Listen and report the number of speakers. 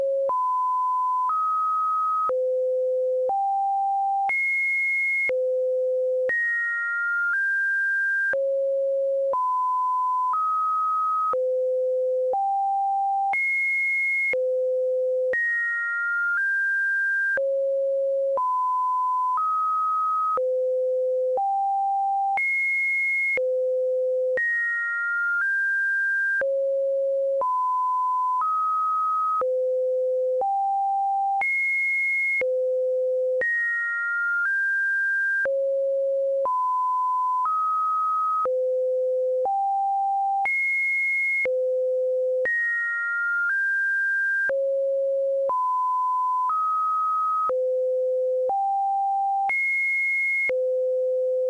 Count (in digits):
0